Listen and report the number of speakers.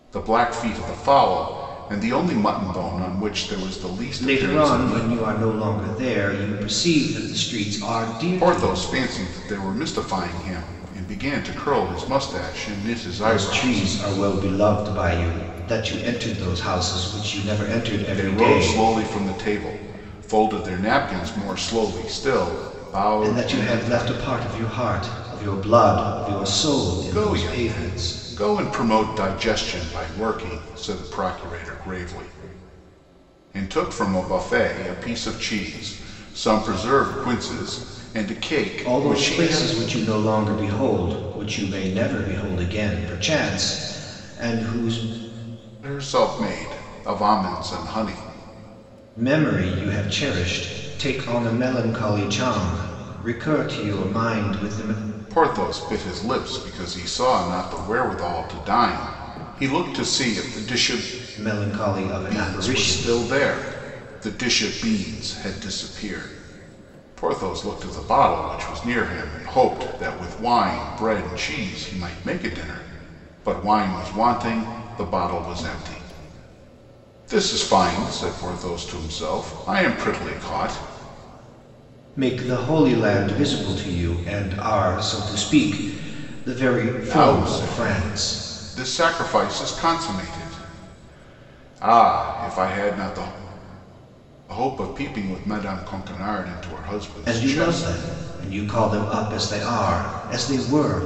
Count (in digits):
2